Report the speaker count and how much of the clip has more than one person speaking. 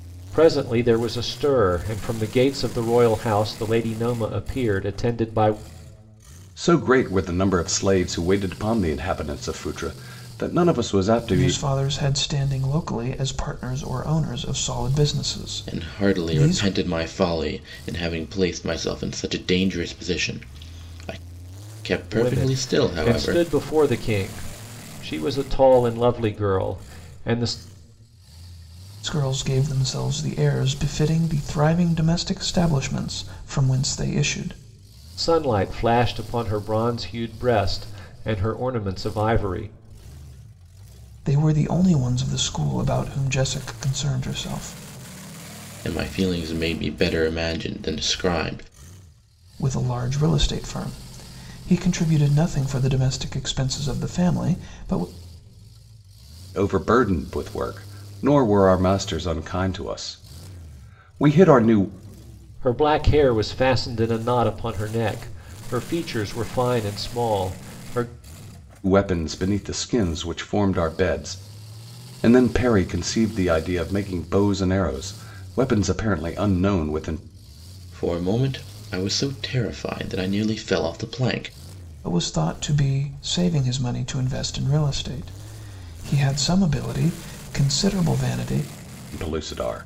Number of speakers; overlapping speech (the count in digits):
4, about 3%